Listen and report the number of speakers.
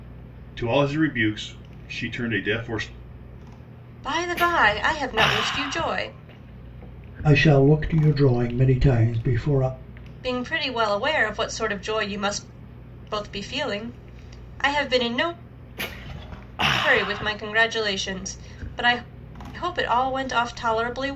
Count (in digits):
3